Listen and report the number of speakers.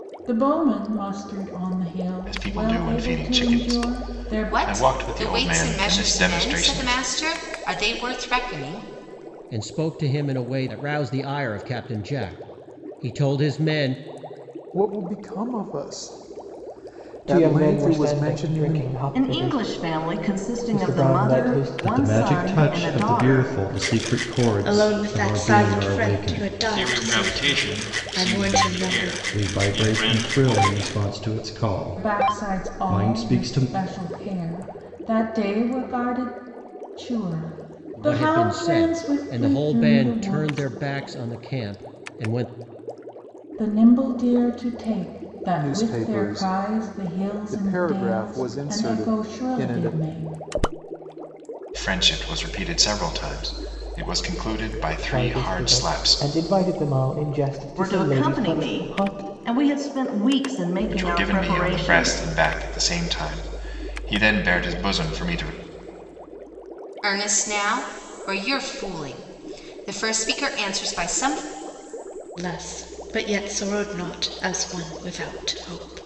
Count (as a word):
ten